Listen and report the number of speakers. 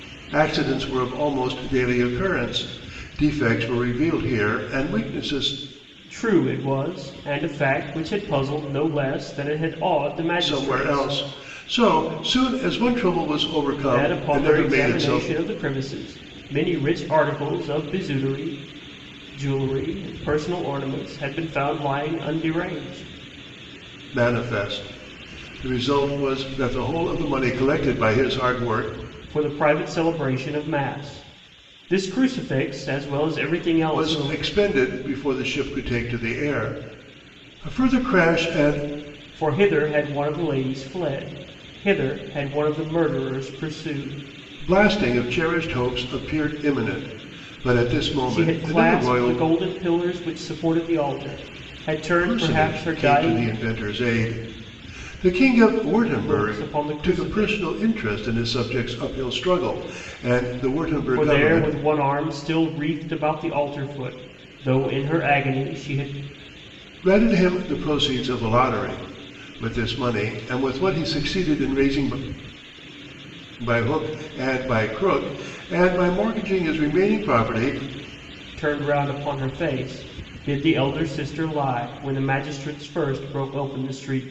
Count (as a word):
two